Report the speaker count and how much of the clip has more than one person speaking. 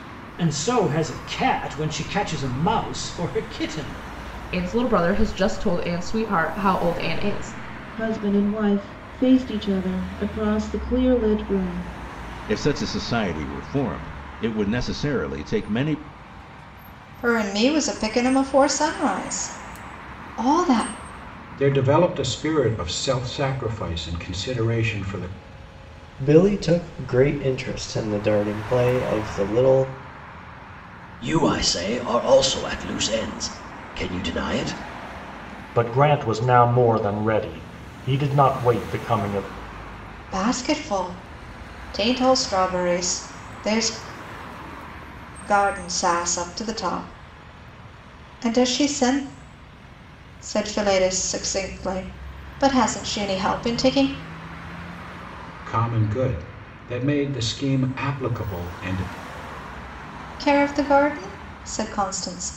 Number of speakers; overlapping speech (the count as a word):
nine, no overlap